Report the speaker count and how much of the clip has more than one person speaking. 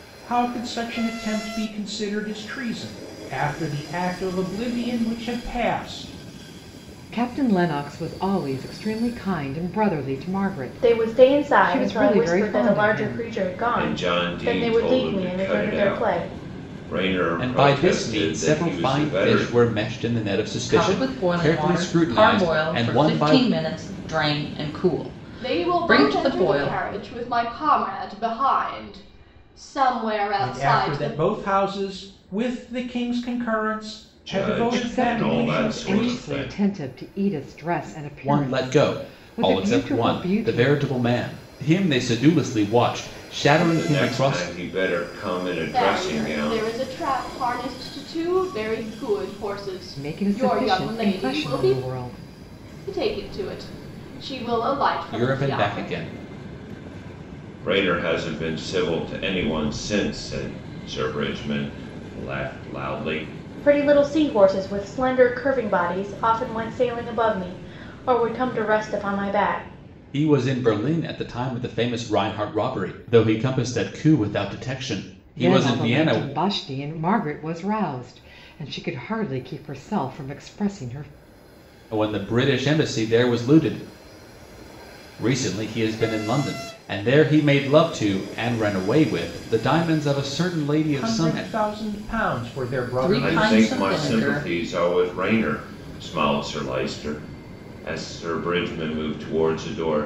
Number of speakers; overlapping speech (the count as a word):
seven, about 25%